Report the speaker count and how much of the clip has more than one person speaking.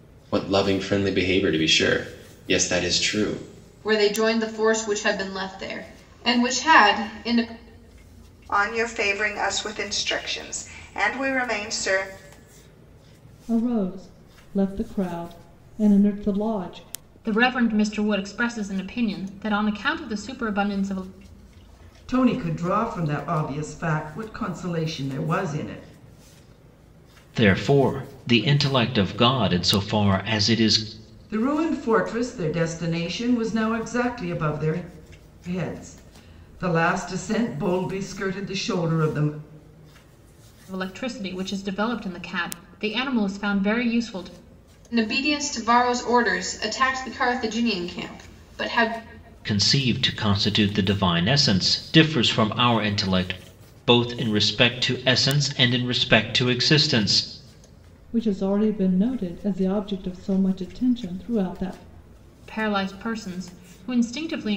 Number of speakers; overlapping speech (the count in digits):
7, no overlap